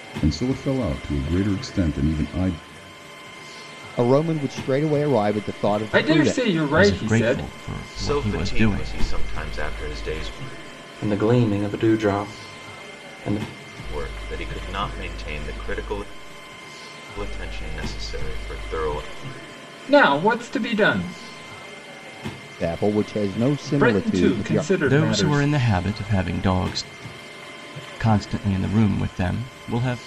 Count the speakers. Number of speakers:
six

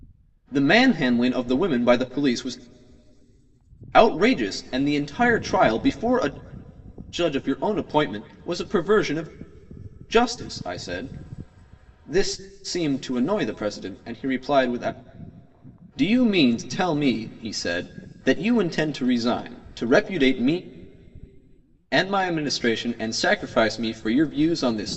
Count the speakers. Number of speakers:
one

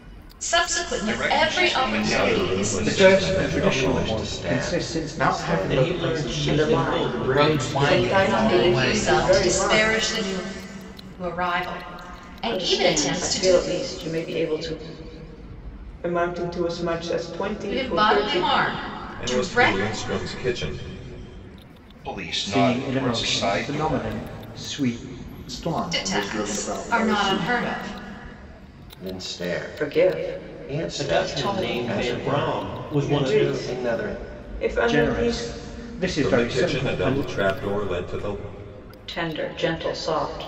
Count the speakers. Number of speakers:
ten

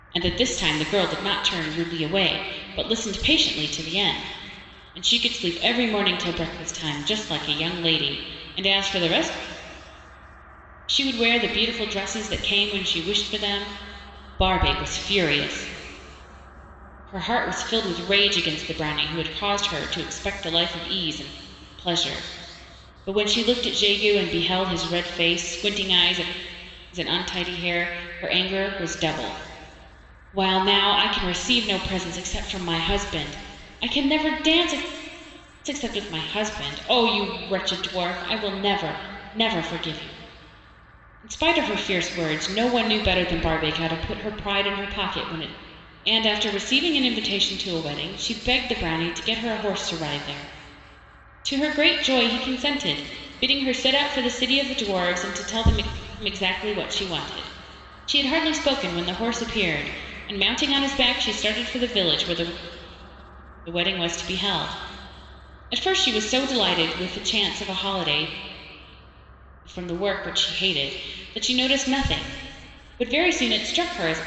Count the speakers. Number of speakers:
one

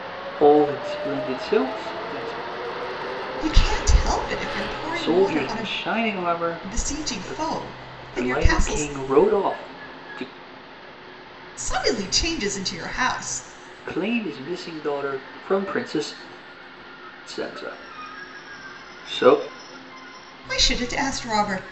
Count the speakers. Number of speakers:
two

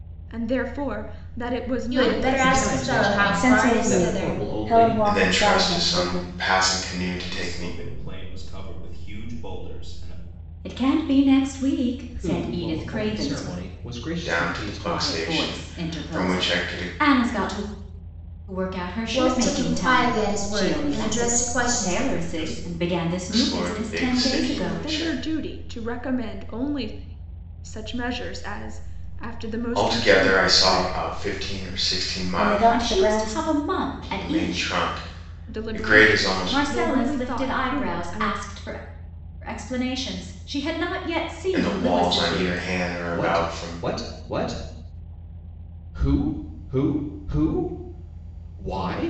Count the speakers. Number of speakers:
seven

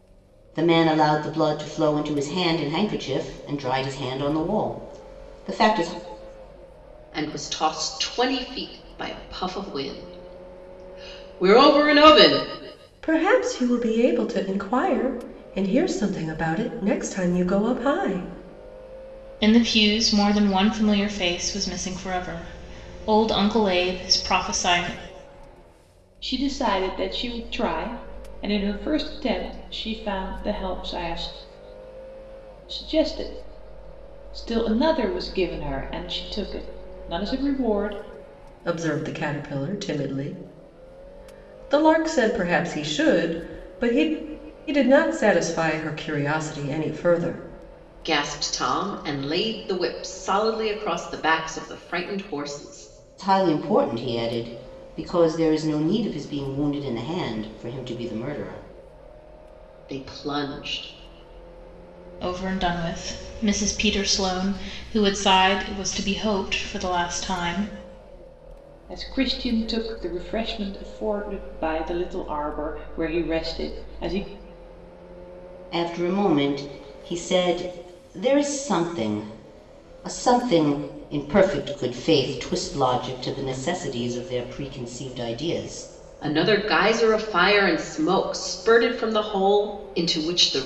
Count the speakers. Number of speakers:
five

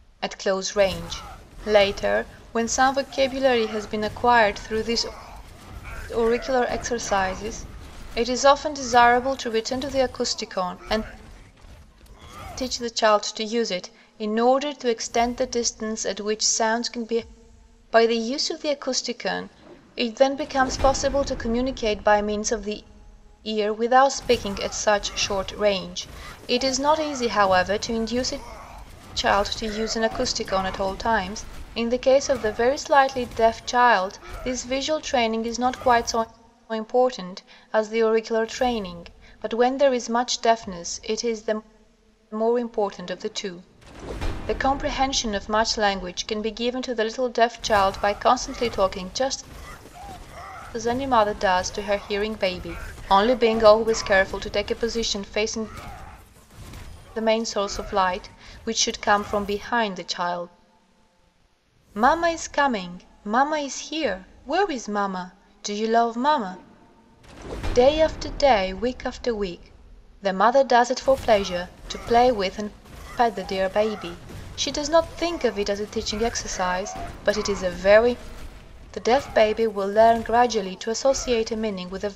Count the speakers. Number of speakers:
one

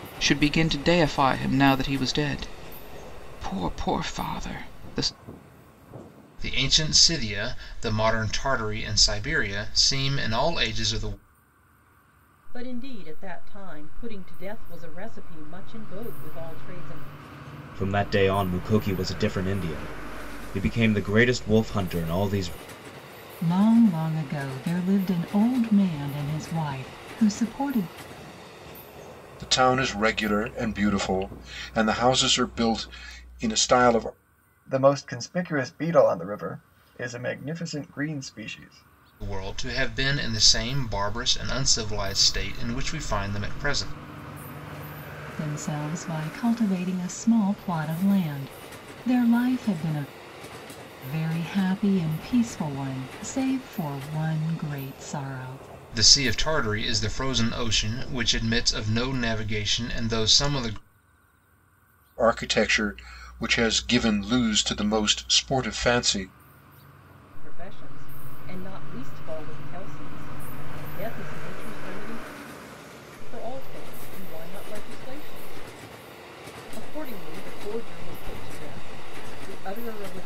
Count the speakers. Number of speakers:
seven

